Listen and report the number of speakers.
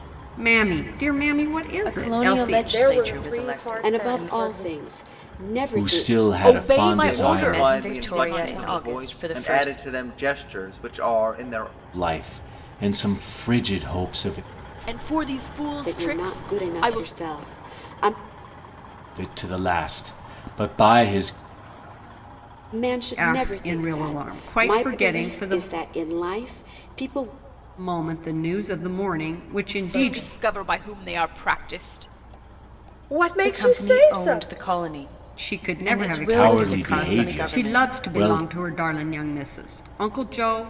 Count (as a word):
seven